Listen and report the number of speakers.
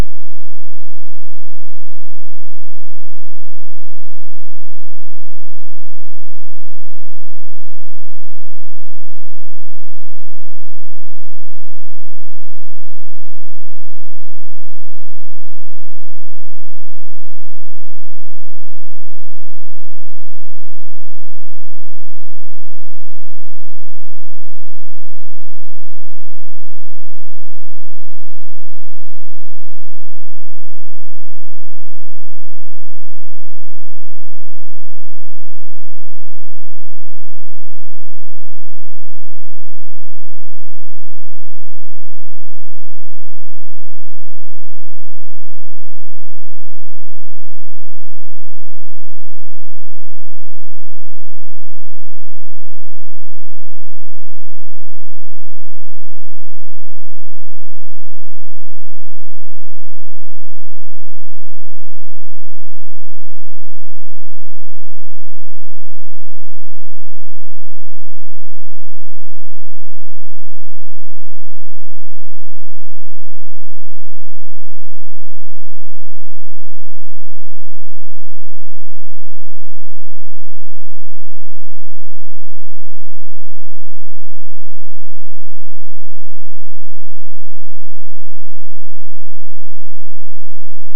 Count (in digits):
0